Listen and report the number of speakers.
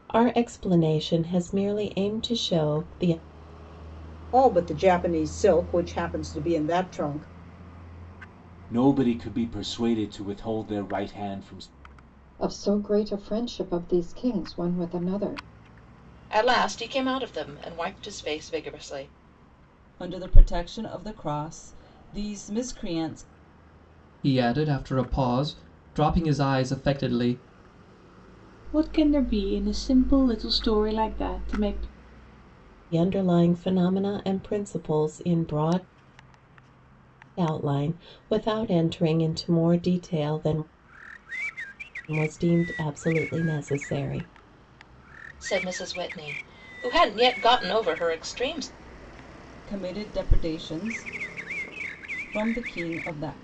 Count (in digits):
8